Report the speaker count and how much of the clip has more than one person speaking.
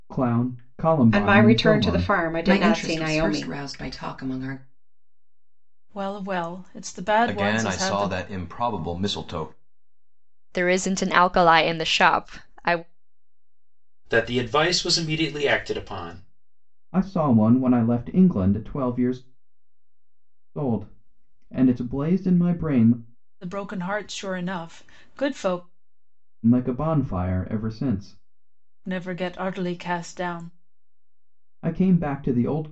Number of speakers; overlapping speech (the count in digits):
7, about 9%